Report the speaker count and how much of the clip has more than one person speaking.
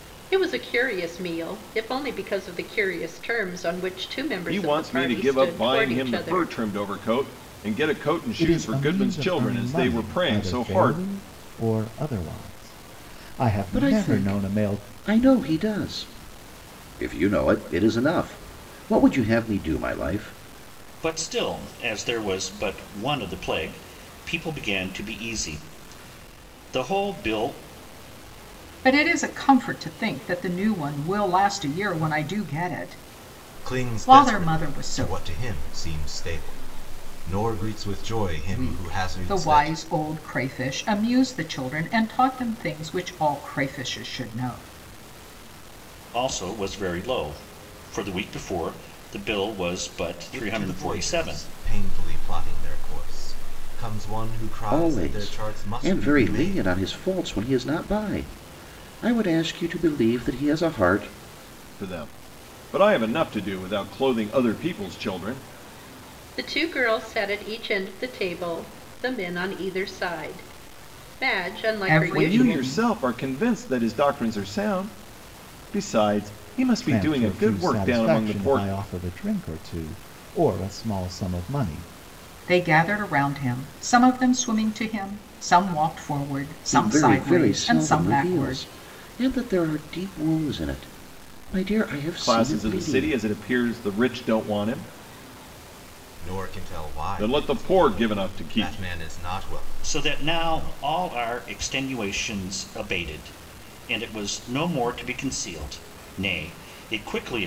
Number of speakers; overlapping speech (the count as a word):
seven, about 20%